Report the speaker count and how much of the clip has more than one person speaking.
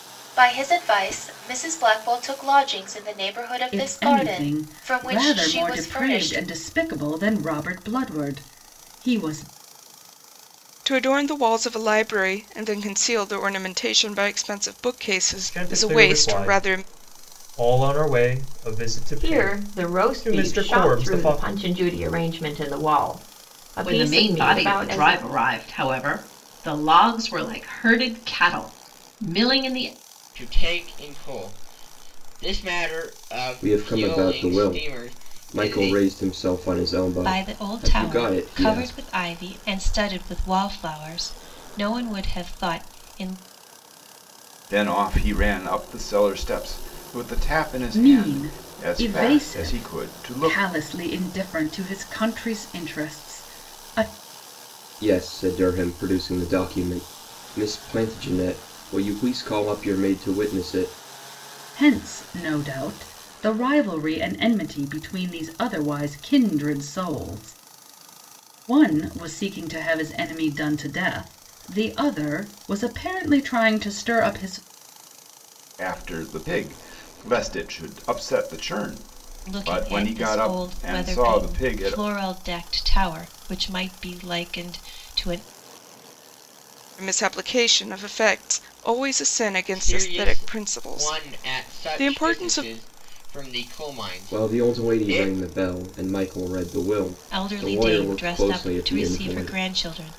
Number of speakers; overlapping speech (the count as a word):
ten, about 24%